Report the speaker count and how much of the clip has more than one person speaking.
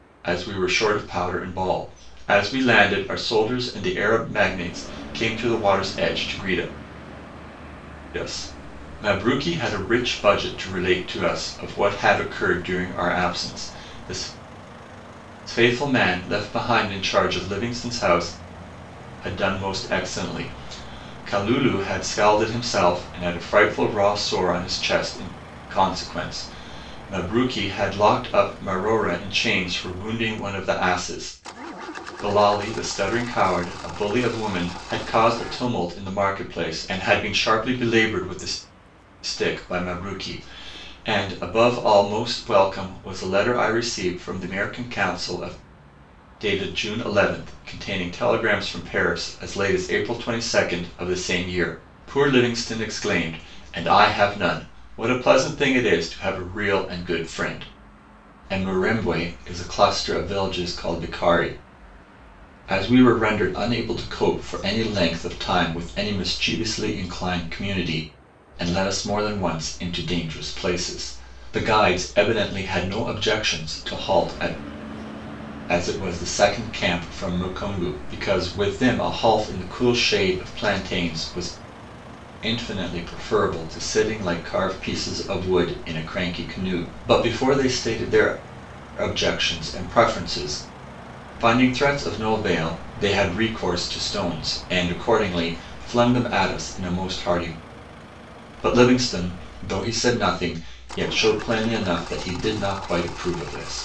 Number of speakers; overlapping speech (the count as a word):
one, no overlap